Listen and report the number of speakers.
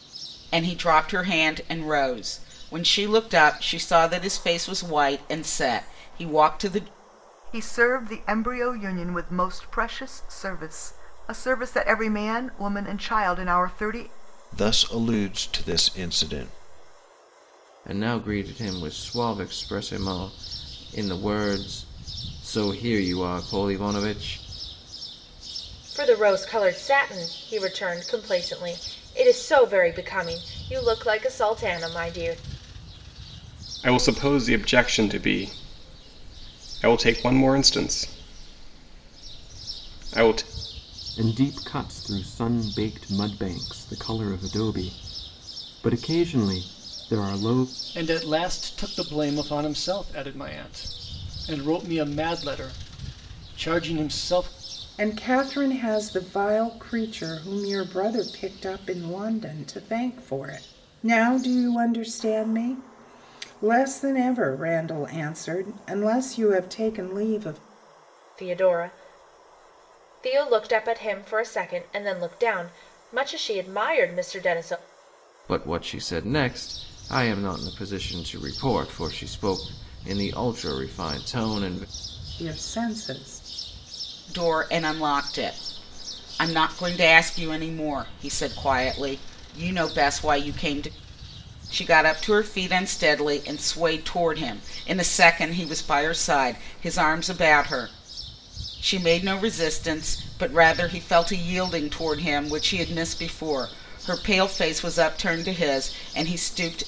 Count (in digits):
9